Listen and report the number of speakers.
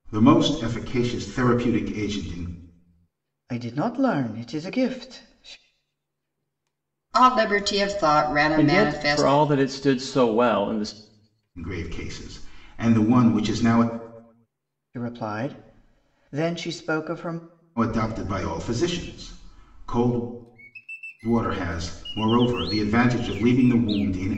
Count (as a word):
four